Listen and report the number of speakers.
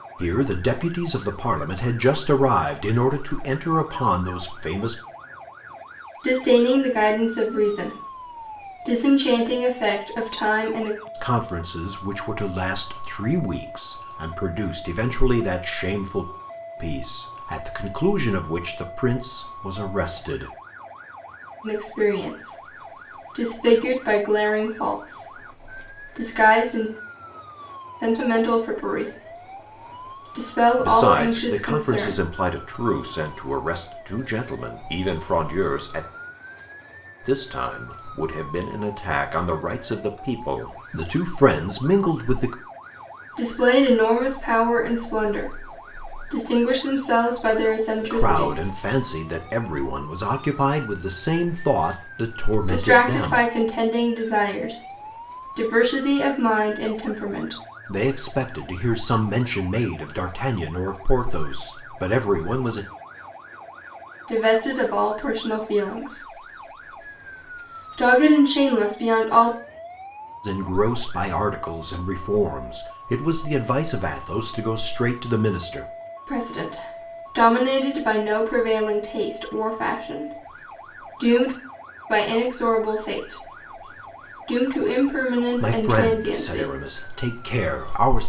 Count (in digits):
2